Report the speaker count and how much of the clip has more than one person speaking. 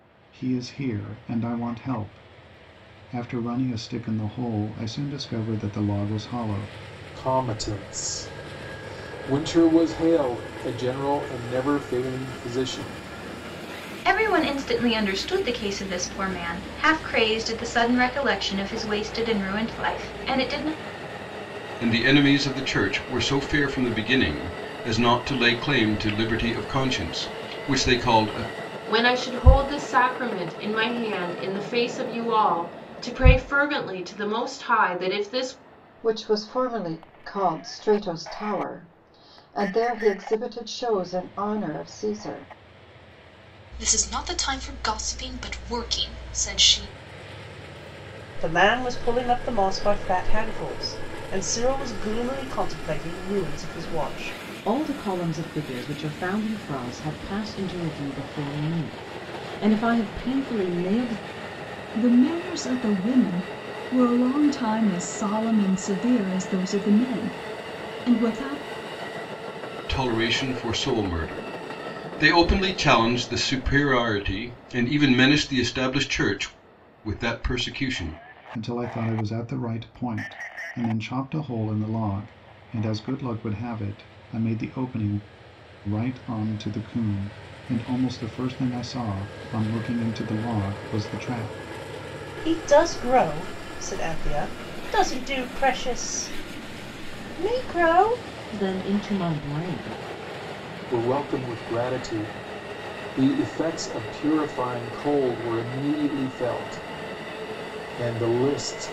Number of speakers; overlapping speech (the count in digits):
10, no overlap